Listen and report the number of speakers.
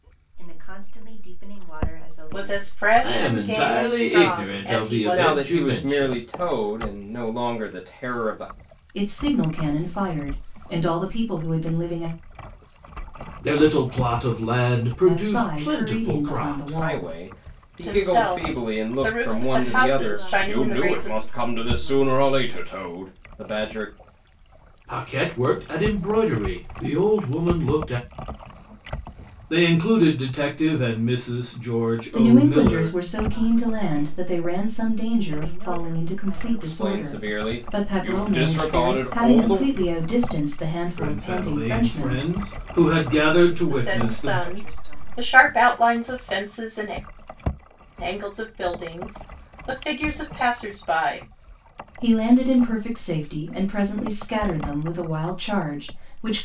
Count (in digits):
5